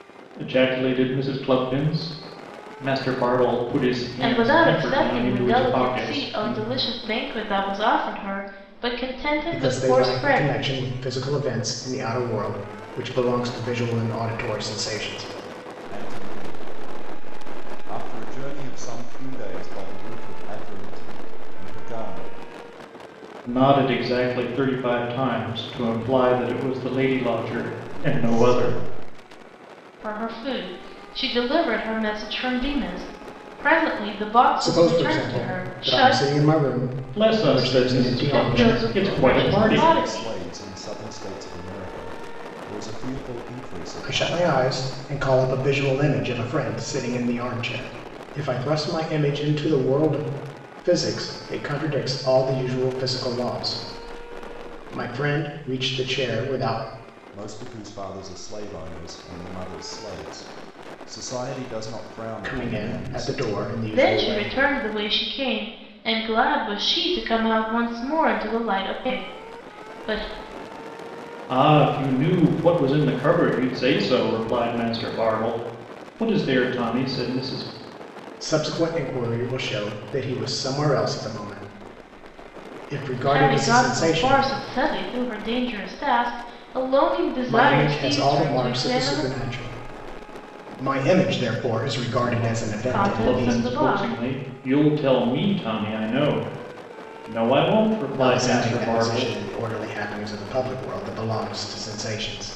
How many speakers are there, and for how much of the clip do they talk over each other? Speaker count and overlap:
four, about 18%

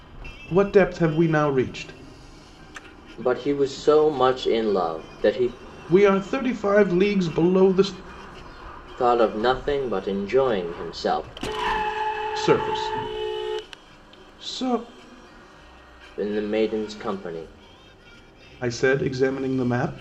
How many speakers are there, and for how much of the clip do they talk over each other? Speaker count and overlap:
two, no overlap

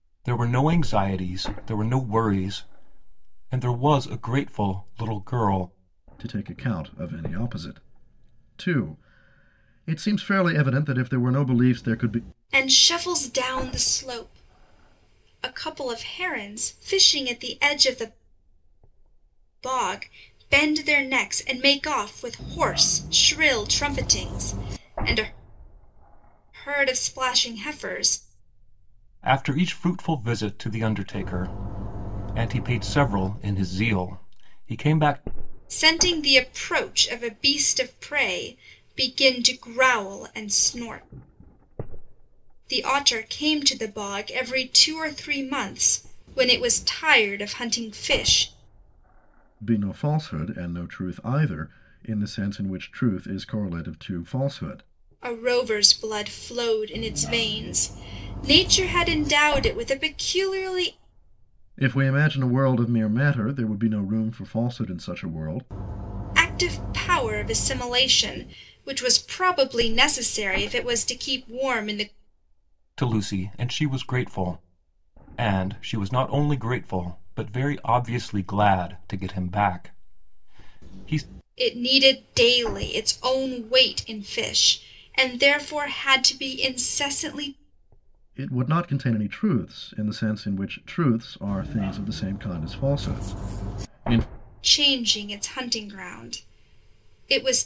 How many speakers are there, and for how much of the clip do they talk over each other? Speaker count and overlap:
three, no overlap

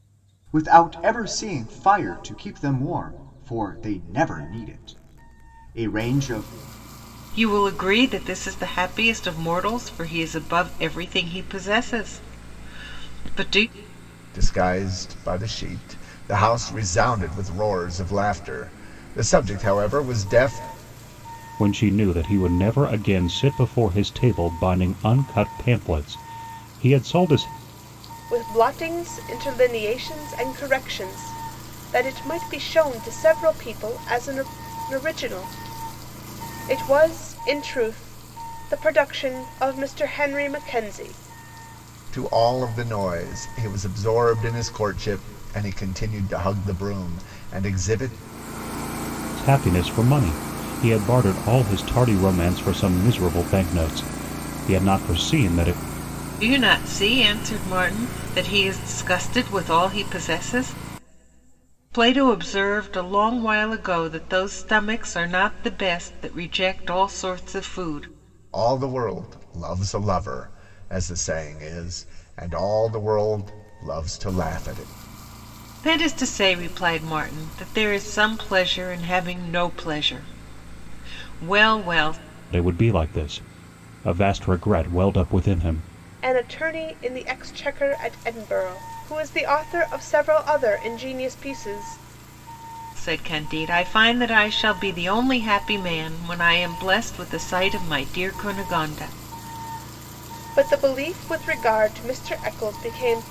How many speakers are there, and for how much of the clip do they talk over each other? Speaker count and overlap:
five, no overlap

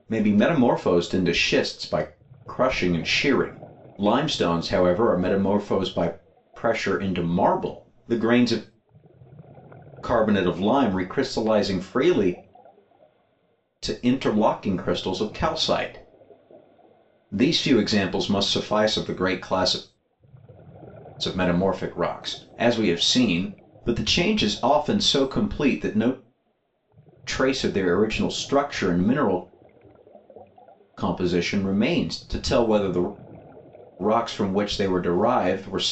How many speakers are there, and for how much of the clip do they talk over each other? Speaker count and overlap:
one, no overlap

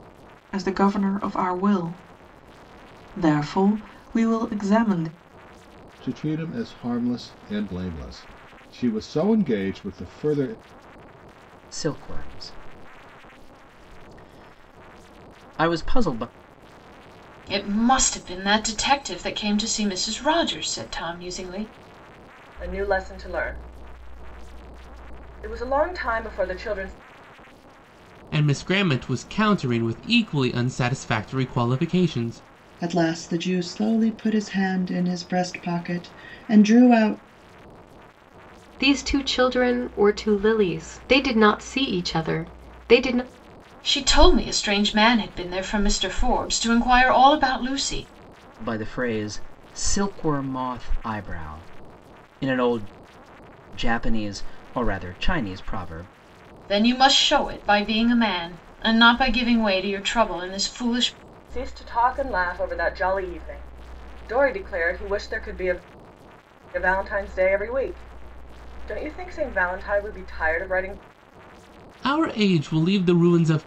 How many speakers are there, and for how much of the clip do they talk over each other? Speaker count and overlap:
eight, no overlap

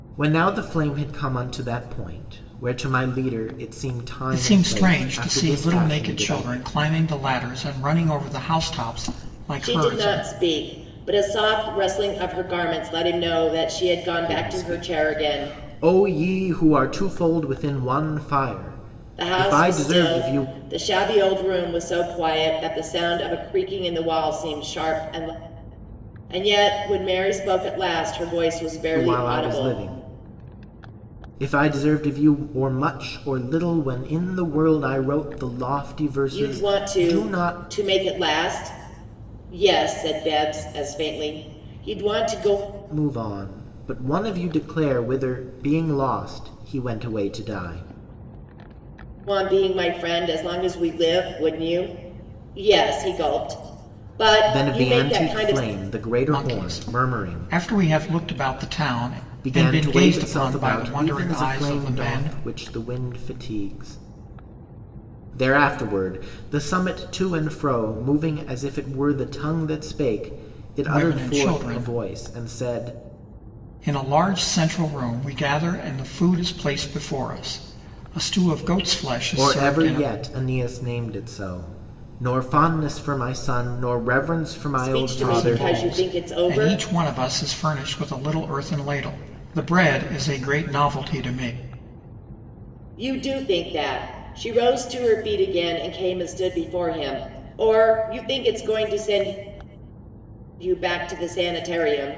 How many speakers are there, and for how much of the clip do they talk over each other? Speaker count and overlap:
three, about 17%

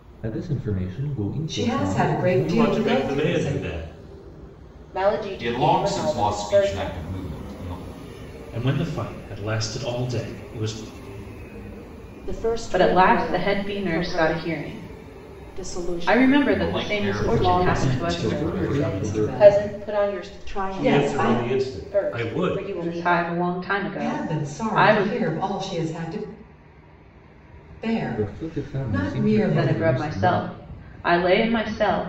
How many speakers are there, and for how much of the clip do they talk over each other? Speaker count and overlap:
eight, about 51%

